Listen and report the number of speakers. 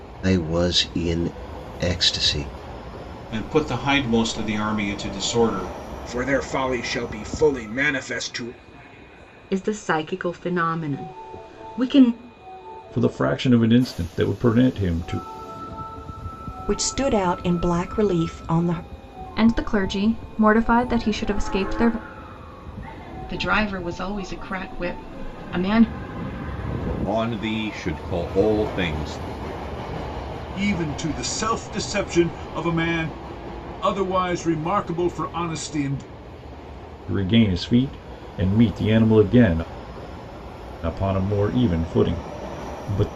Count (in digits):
10